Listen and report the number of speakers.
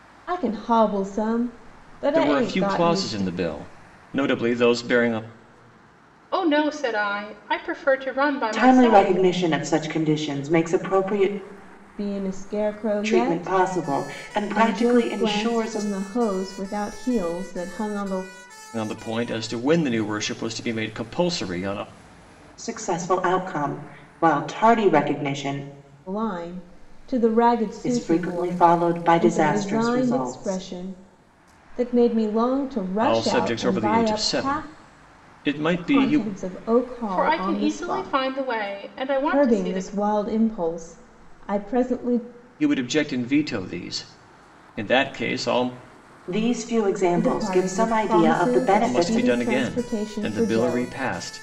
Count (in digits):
4